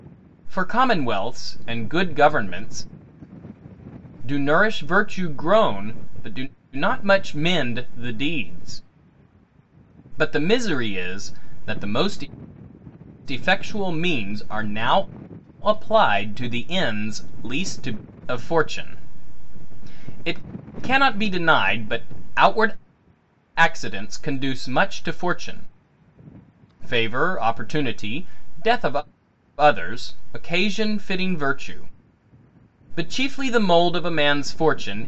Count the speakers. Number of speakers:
1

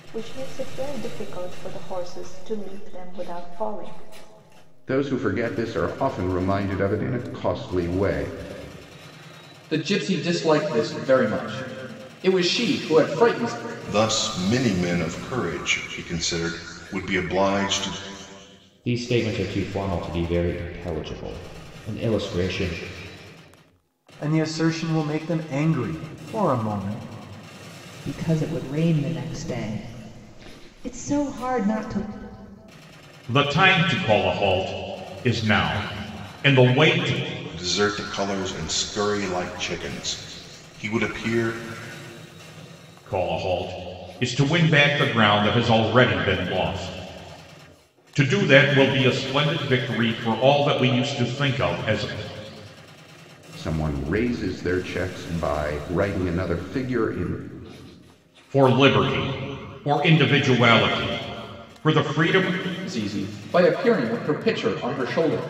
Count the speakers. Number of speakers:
8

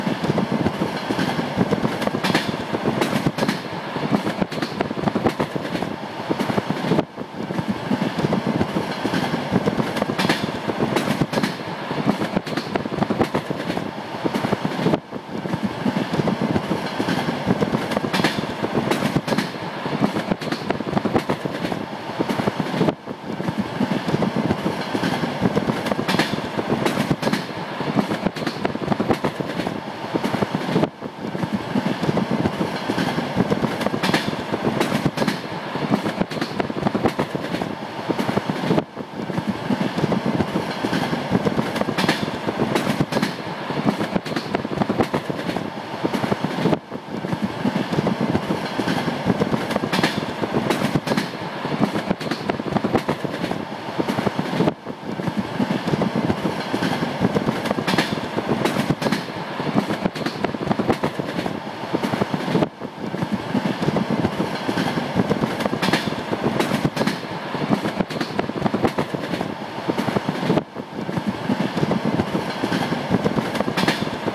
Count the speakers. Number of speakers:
0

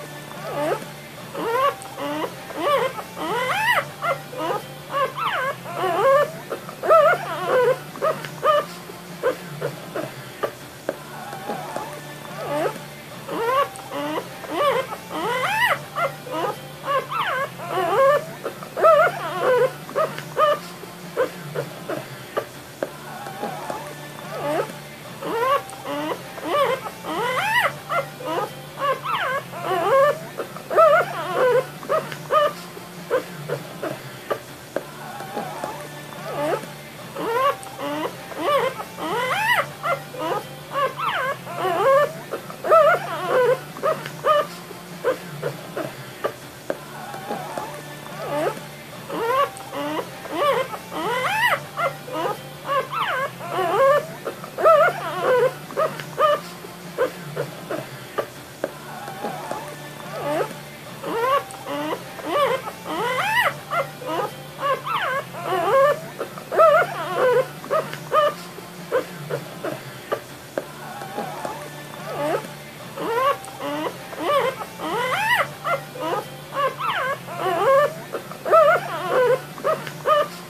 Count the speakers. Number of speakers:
0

